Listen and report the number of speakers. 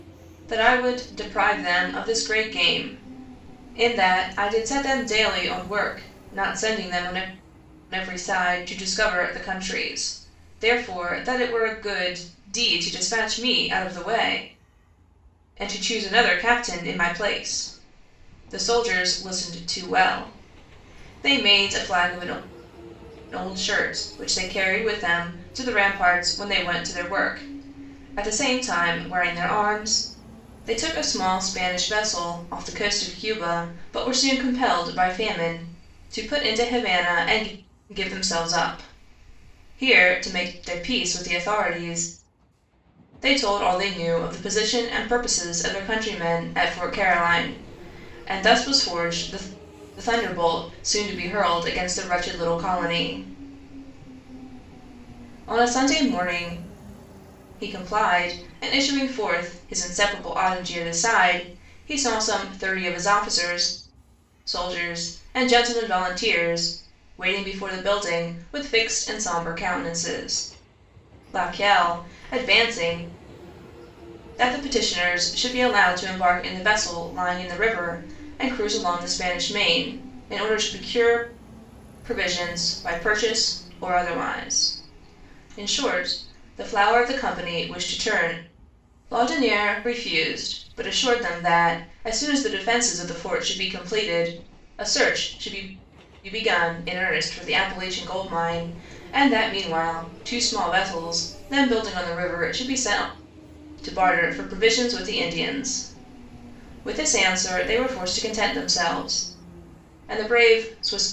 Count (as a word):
one